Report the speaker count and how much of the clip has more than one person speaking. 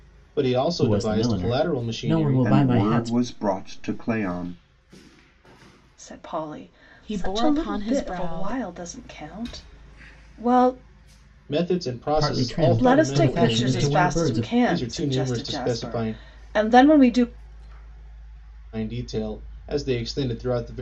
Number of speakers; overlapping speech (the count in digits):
5, about 39%